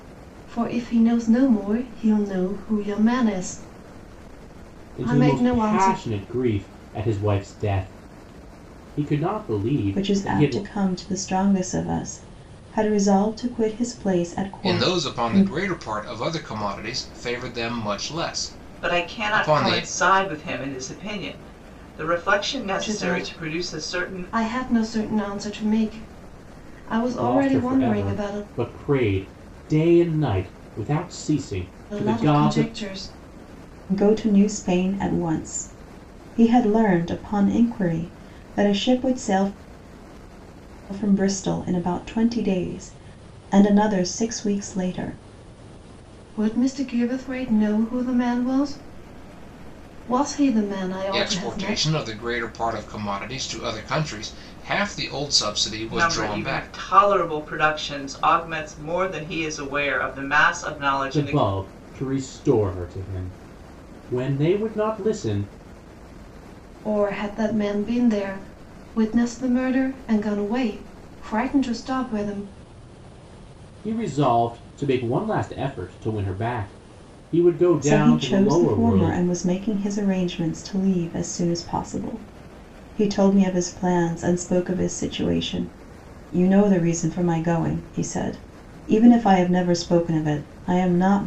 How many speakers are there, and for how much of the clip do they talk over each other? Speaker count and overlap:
5, about 12%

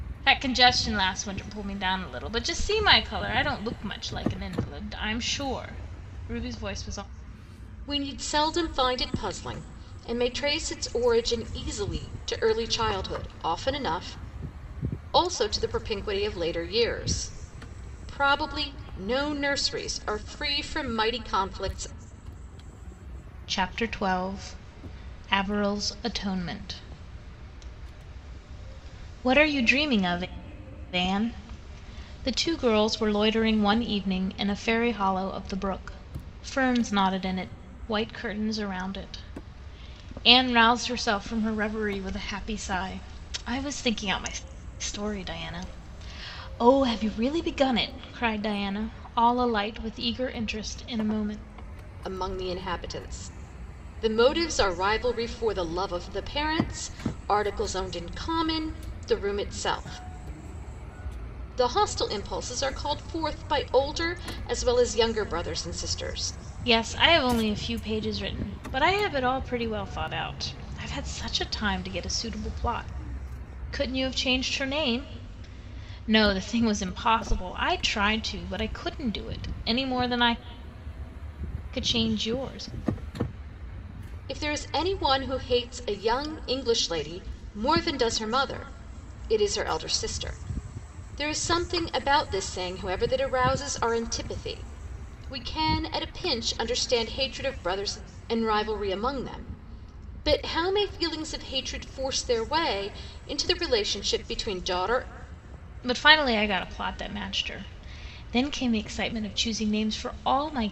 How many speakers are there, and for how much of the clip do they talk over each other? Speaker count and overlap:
2, no overlap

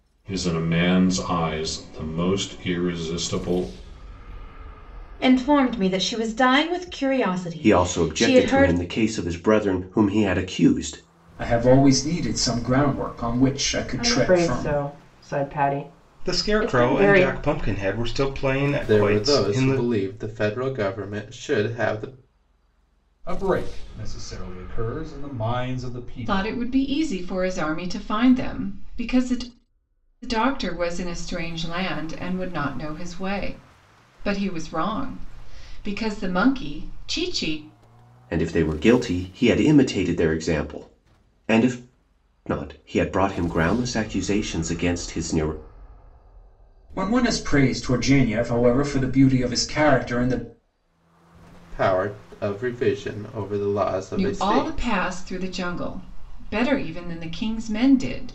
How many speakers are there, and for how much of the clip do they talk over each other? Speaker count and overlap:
9, about 9%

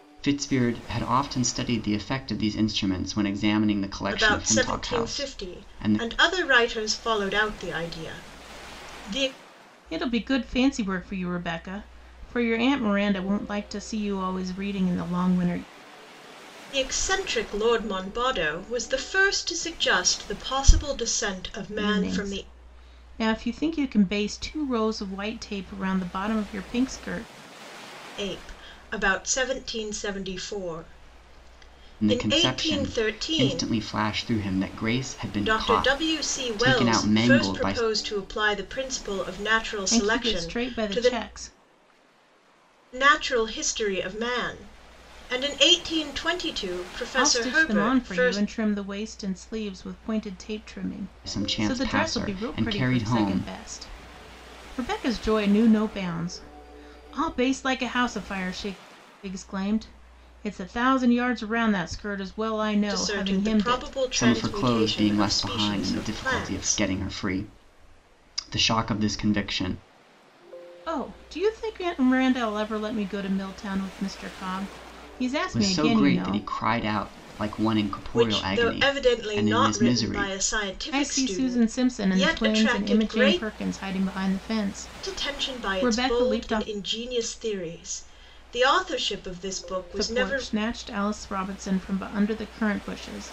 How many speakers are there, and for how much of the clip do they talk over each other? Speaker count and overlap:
3, about 25%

